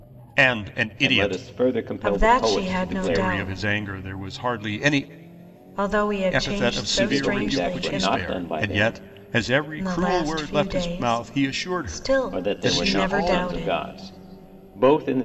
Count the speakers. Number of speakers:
3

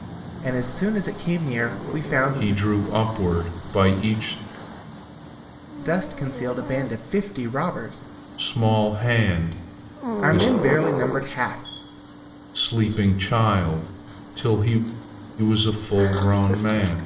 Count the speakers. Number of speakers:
2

